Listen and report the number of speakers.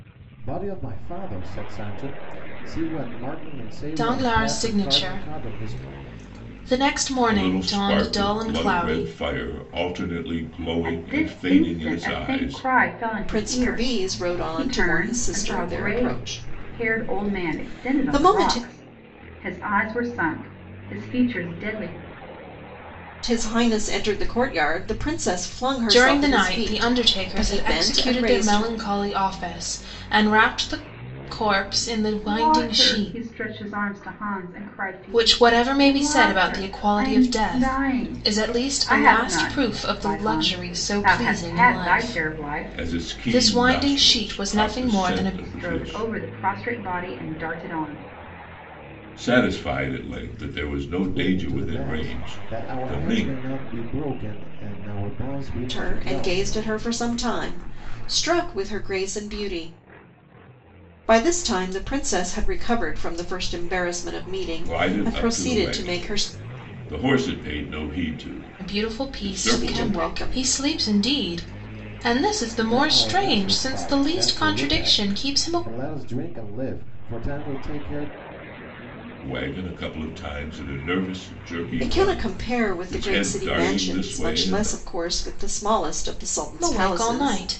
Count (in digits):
5